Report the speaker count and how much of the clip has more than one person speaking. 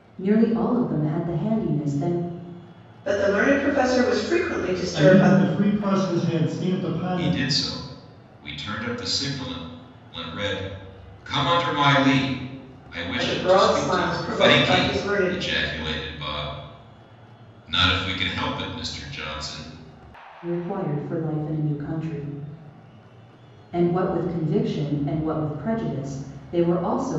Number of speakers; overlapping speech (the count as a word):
four, about 11%